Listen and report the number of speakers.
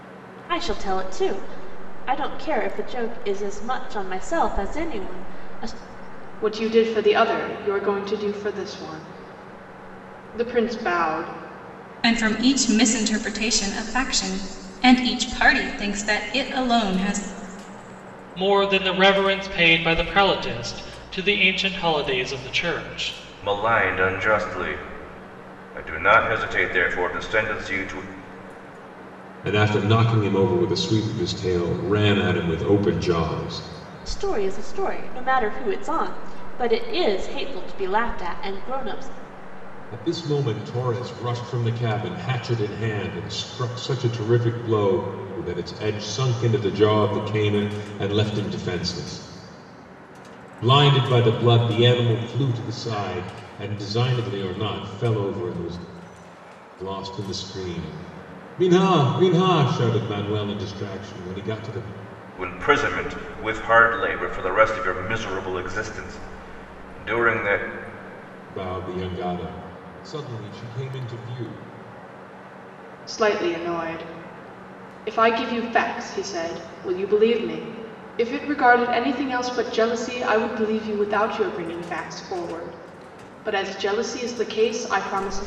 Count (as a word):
six